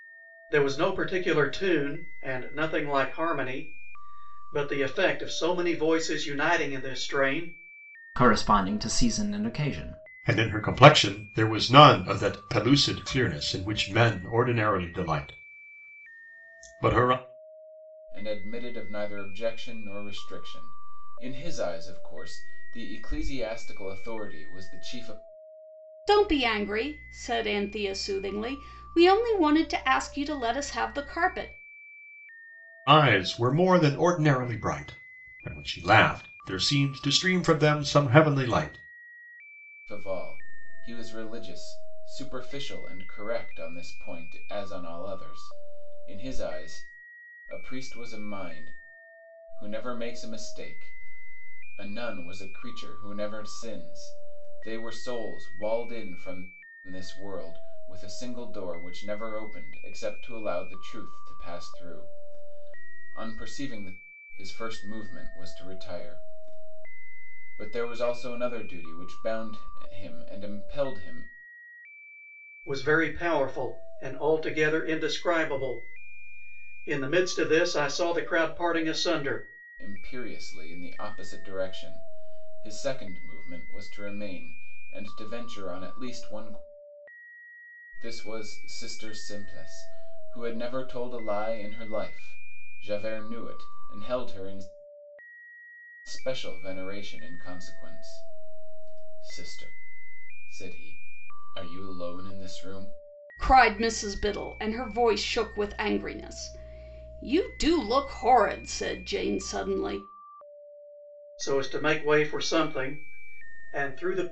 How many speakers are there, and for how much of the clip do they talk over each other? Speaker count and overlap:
five, no overlap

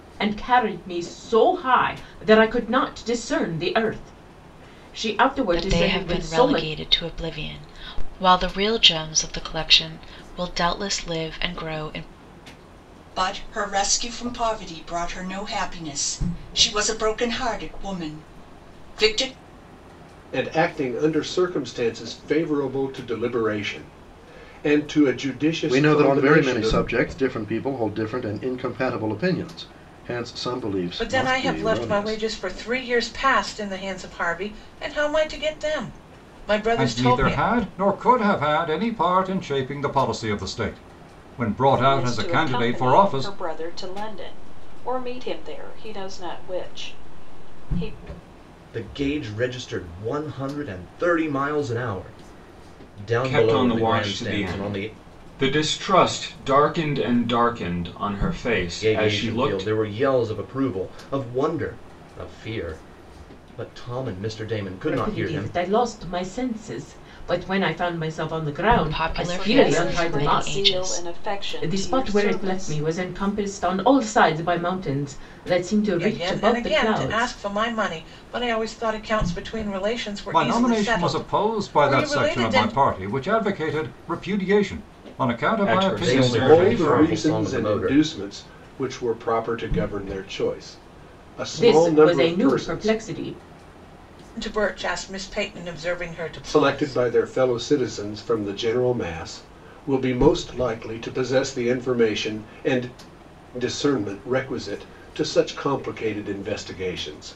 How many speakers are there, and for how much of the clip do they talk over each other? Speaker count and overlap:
ten, about 20%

